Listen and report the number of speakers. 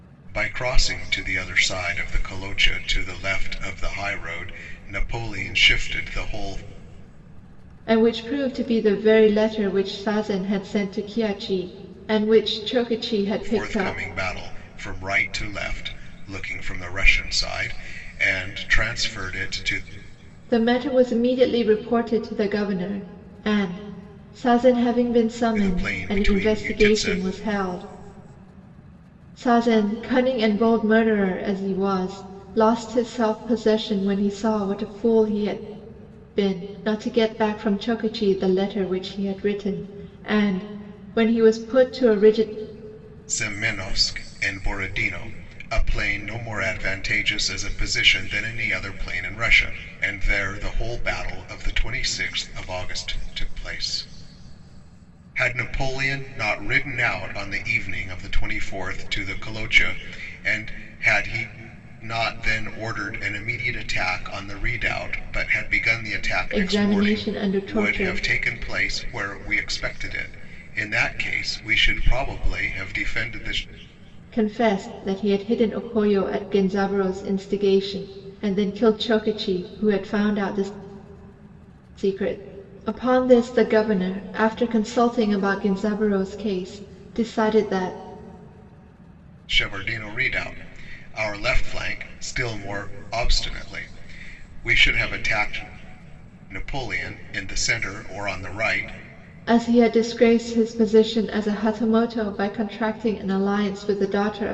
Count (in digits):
2